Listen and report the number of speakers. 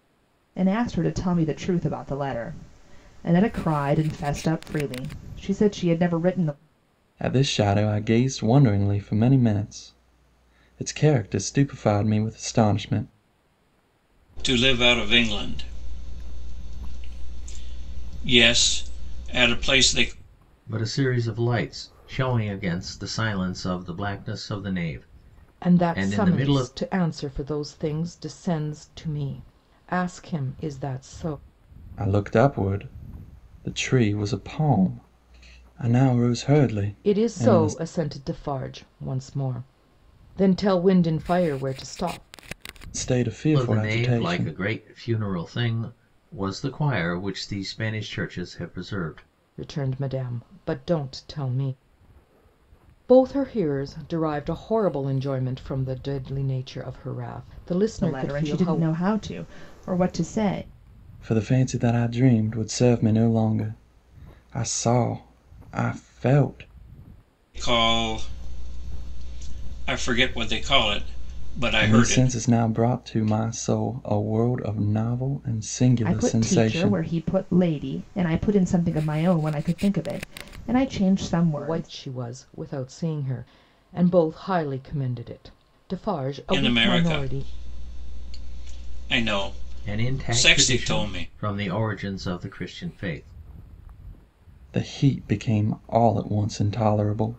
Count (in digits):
5